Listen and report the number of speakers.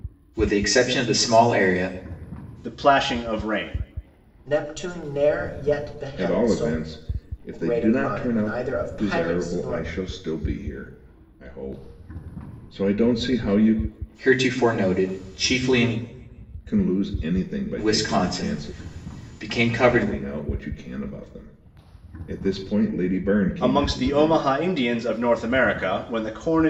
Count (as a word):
four